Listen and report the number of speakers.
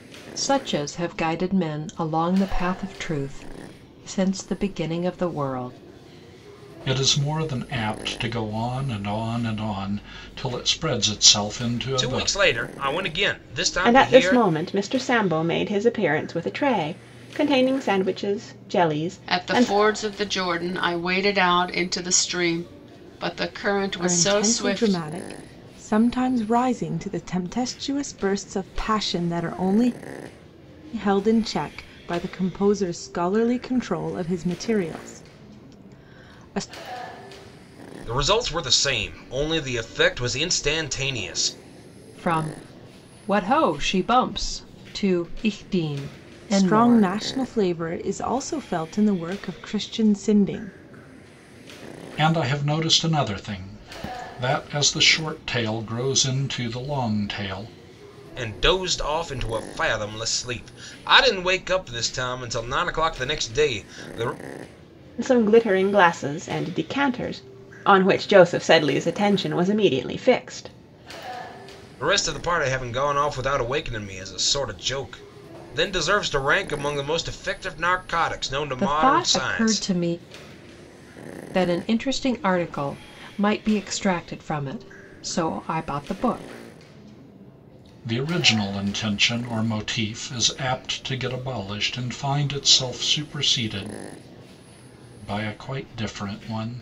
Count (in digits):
6